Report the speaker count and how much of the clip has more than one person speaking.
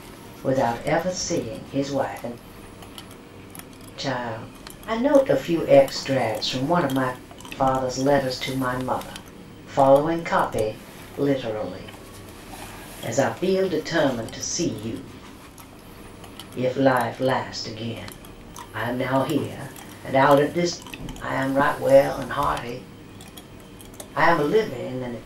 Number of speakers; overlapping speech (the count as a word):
one, no overlap